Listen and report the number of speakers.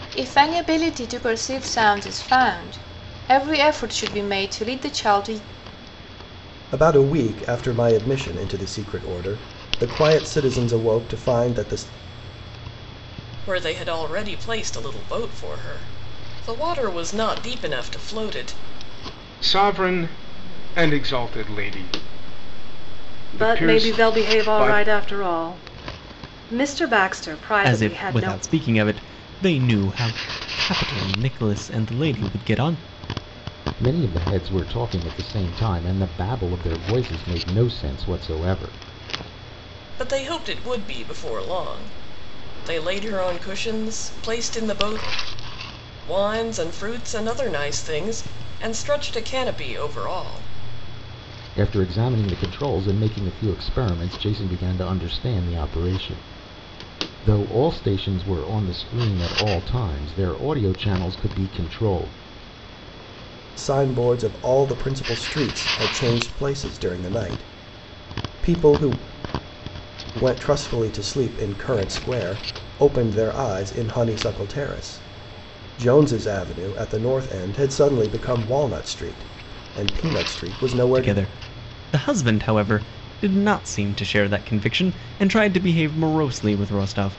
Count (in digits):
7